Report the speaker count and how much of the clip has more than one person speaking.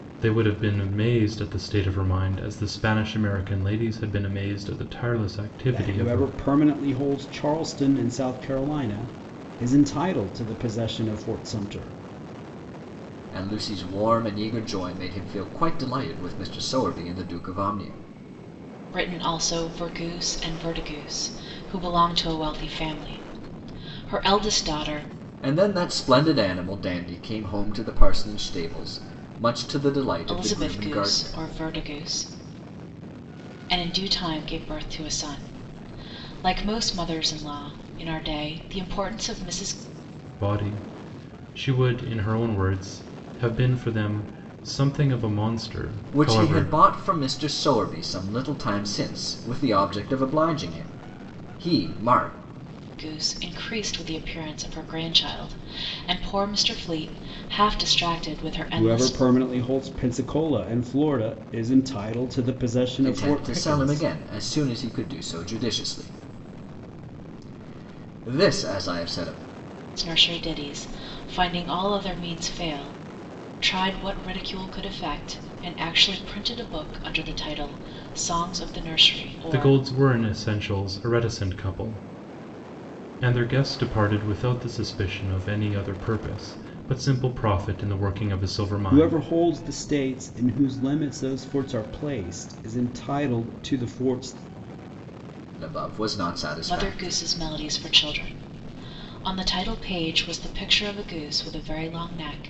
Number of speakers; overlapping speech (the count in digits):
4, about 5%